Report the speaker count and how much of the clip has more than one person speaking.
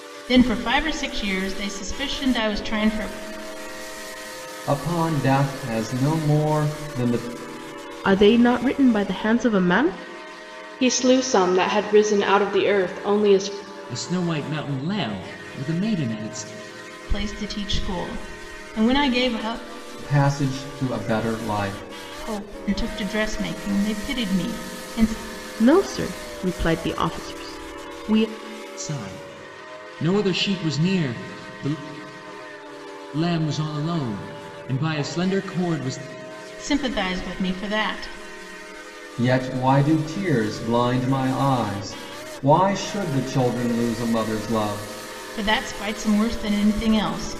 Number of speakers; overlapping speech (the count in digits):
5, no overlap